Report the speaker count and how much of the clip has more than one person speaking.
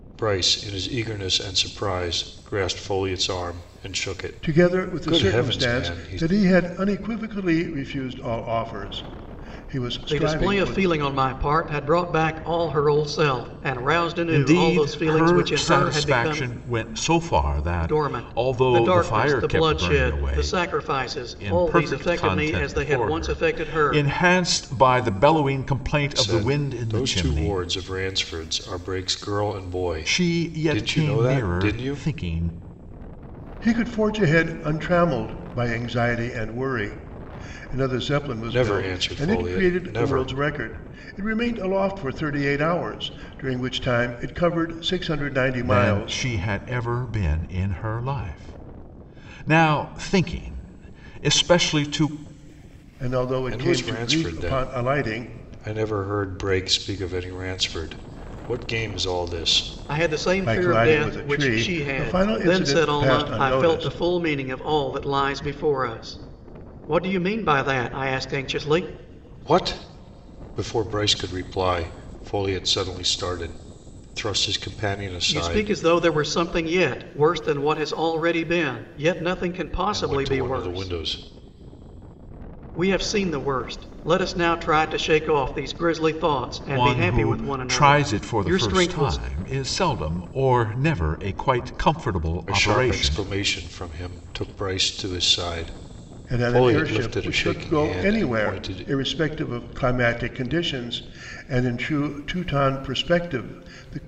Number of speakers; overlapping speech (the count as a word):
four, about 28%